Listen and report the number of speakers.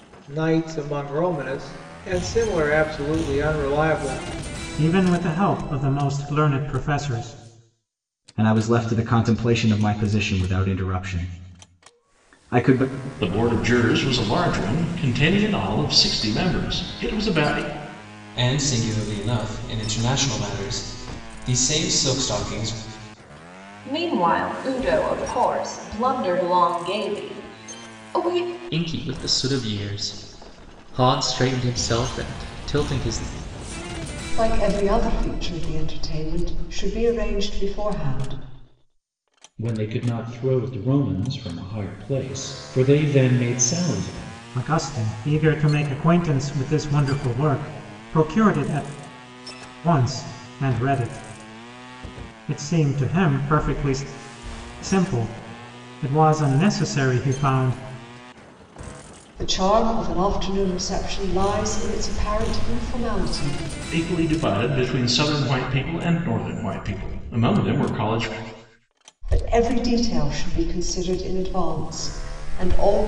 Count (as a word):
nine